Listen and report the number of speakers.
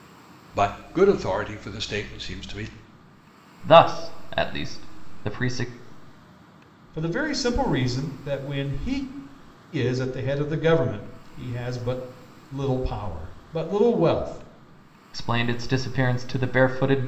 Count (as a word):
three